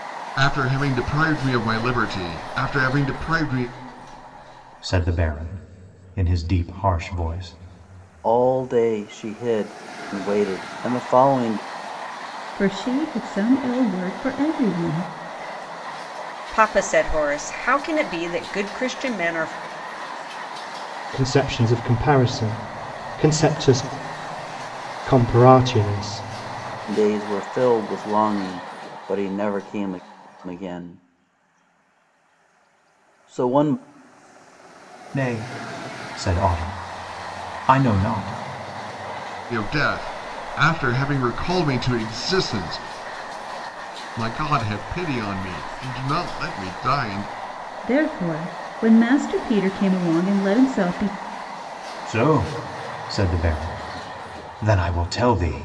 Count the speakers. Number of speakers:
six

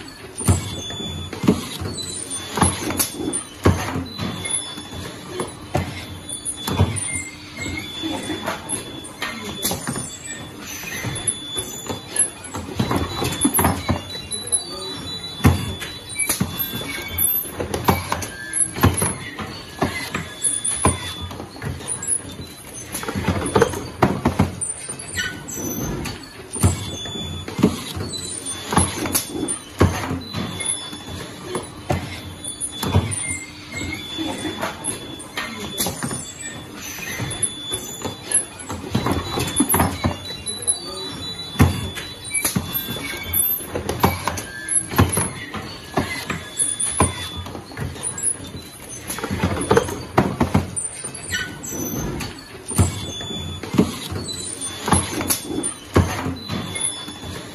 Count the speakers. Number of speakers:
zero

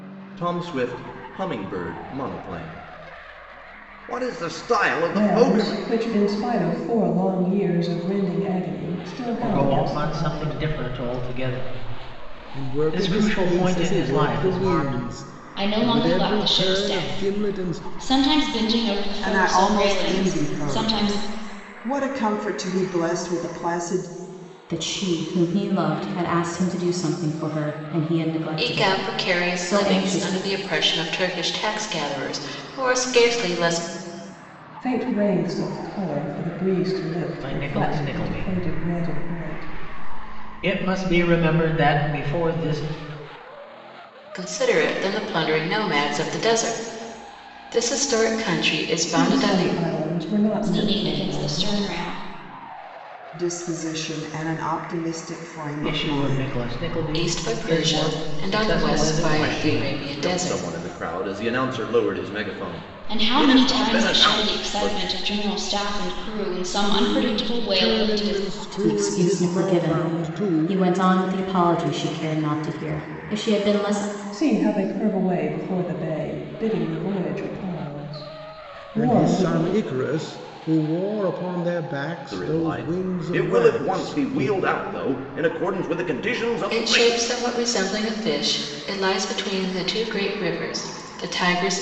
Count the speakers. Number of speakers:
eight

